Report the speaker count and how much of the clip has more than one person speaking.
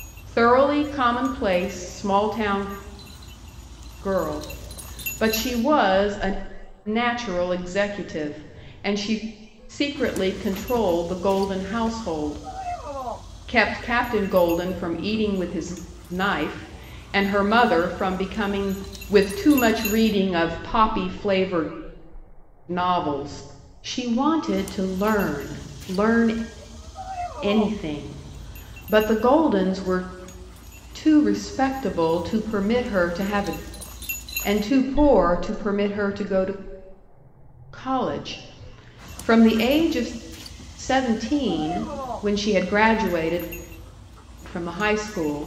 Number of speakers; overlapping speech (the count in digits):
1, no overlap